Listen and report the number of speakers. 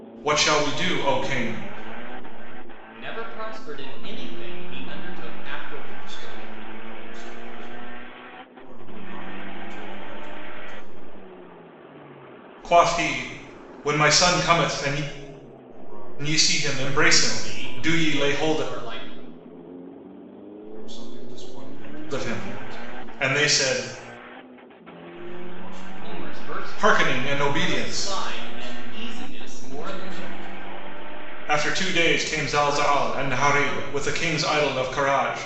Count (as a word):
three